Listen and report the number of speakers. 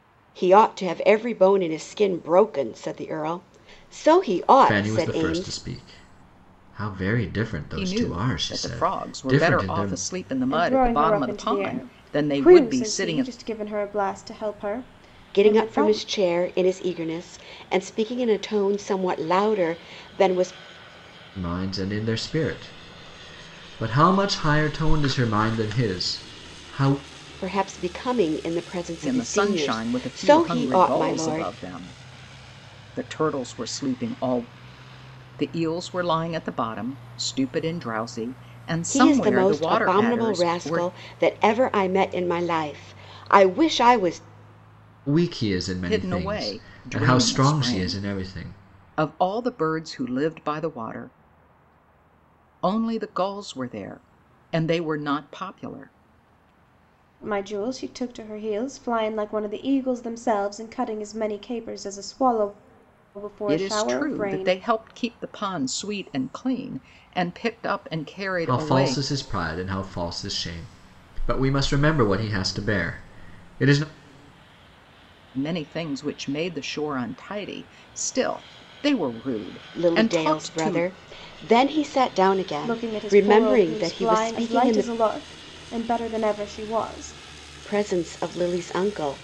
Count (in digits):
4